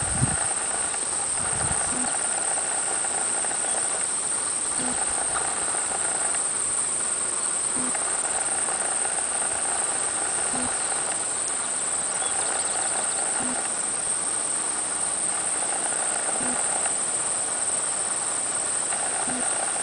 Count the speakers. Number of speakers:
zero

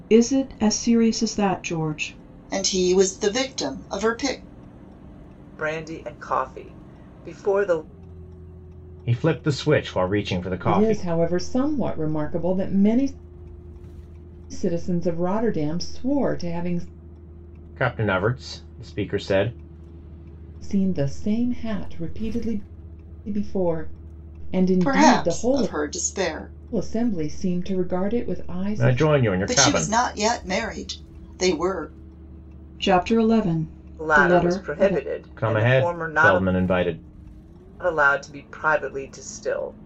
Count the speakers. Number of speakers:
five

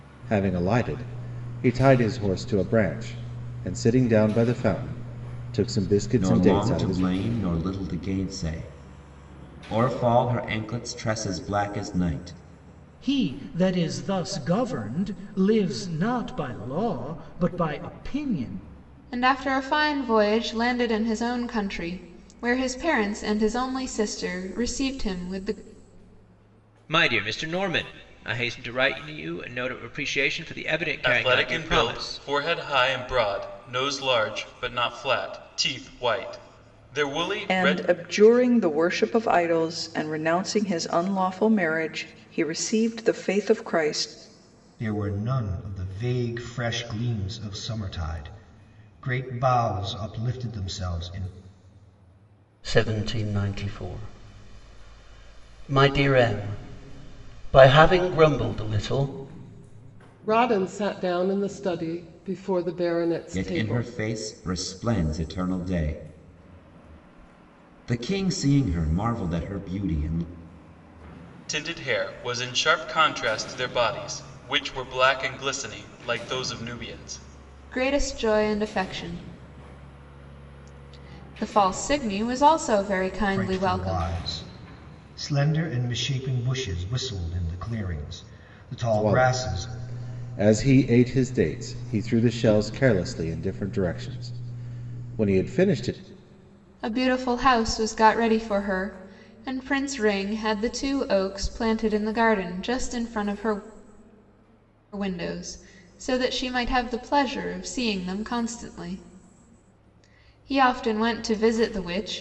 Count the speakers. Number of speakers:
ten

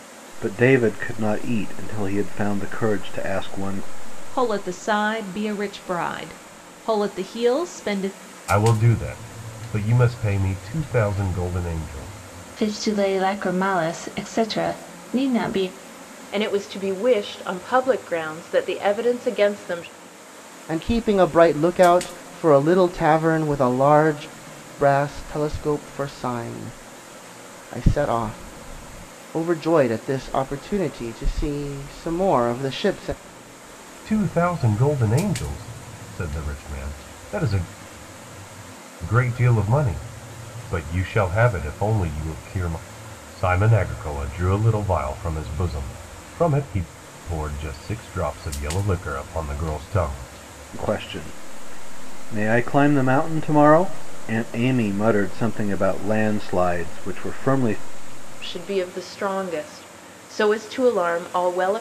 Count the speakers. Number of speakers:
six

